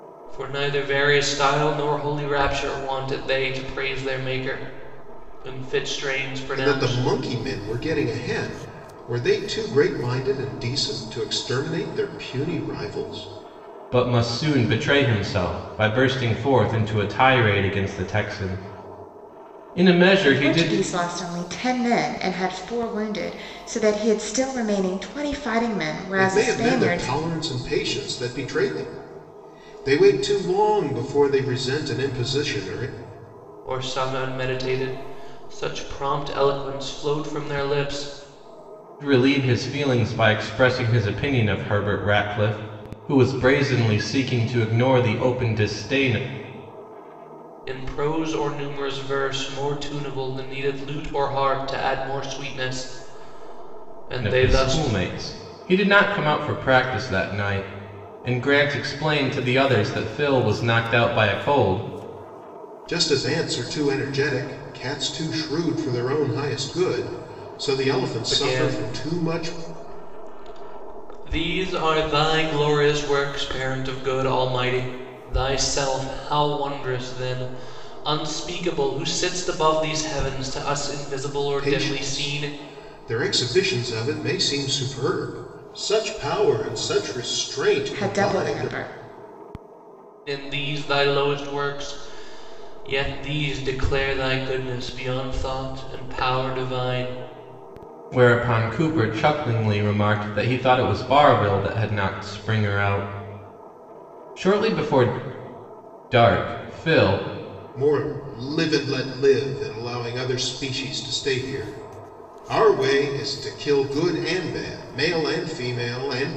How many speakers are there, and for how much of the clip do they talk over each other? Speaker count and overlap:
four, about 5%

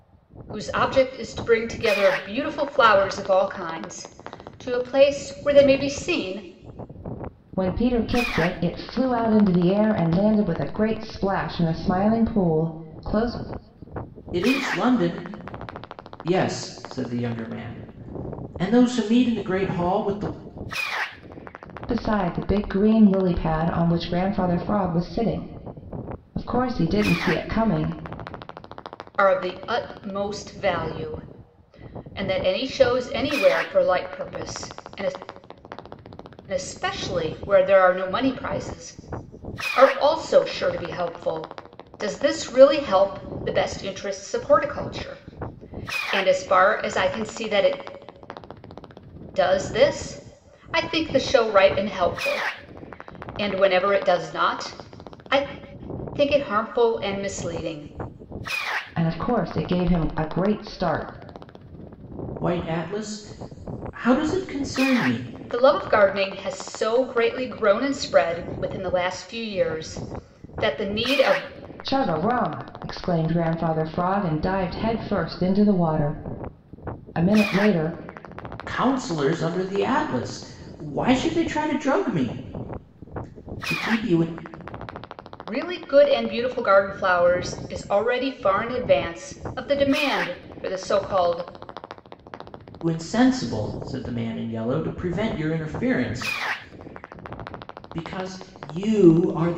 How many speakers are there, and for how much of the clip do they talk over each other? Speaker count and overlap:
three, no overlap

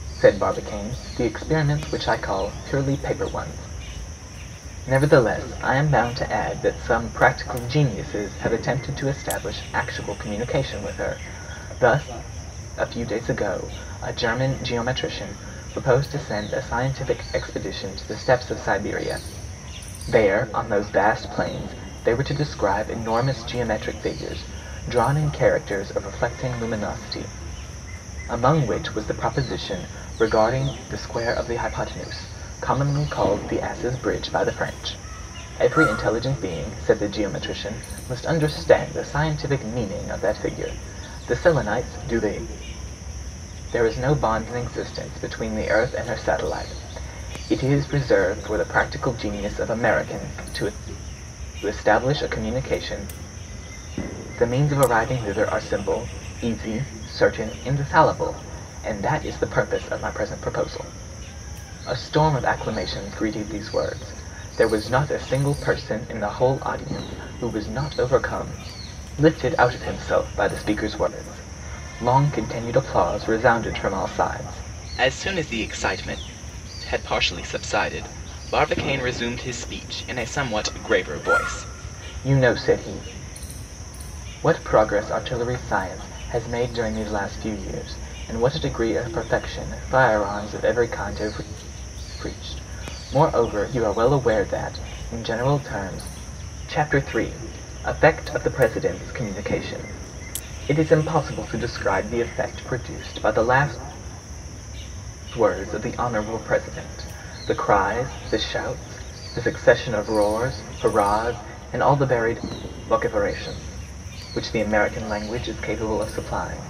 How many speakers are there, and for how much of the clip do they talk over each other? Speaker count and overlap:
one, no overlap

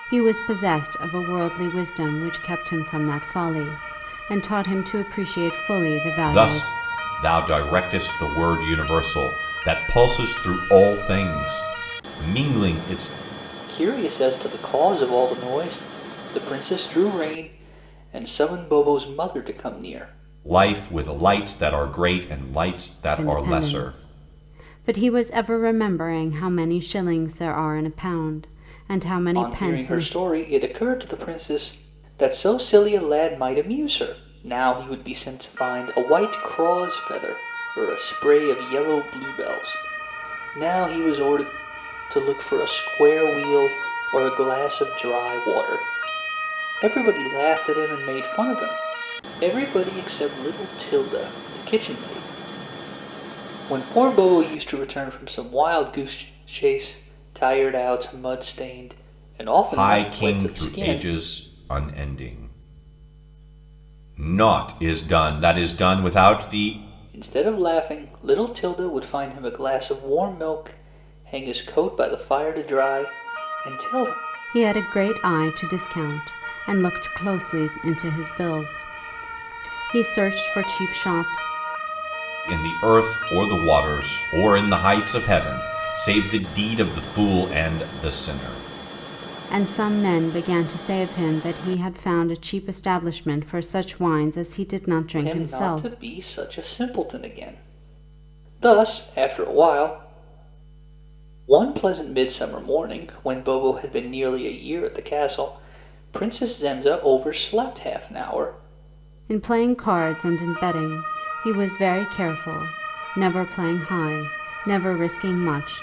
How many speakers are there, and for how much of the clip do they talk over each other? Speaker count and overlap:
three, about 4%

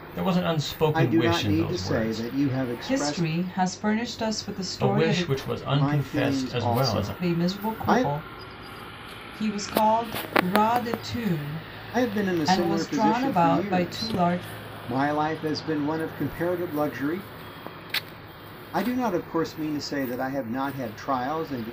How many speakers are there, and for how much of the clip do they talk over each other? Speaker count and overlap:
three, about 30%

